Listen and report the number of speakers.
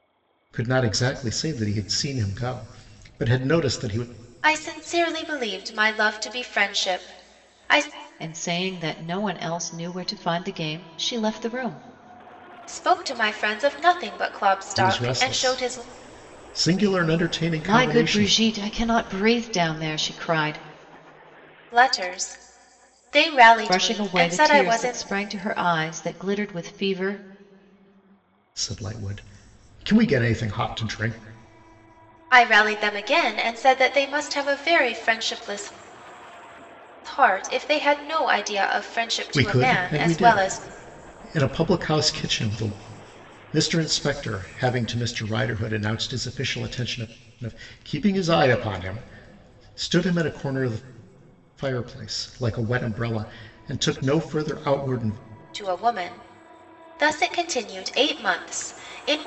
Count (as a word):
three